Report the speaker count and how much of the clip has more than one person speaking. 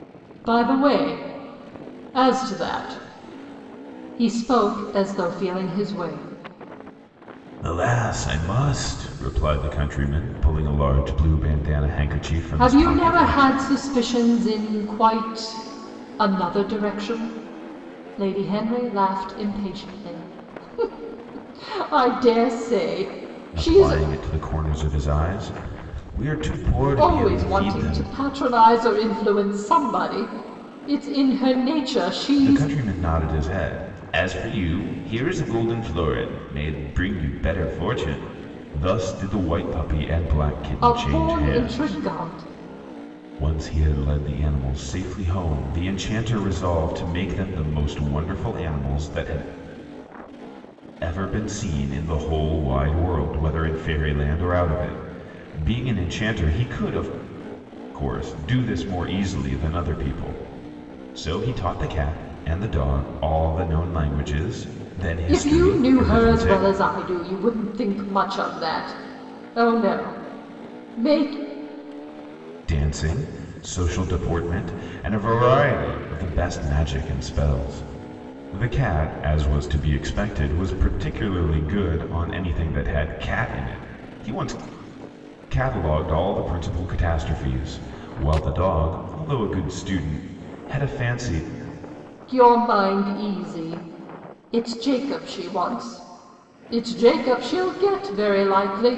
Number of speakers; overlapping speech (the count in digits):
2, about 6%